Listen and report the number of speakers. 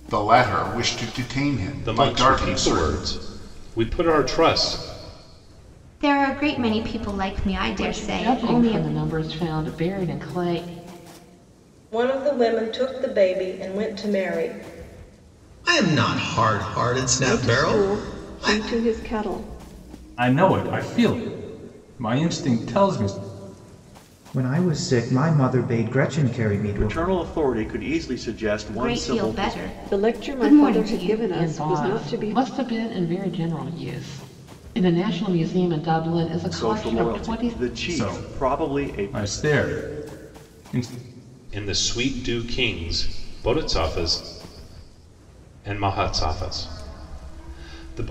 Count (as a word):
ten